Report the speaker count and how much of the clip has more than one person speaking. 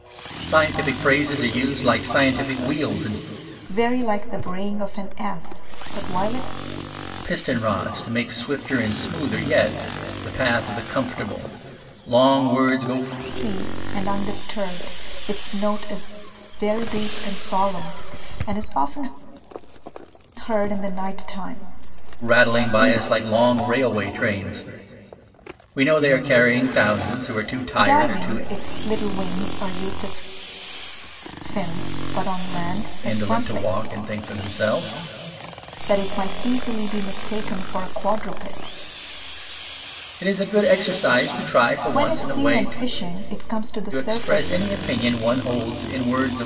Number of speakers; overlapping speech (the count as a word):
two, about 9%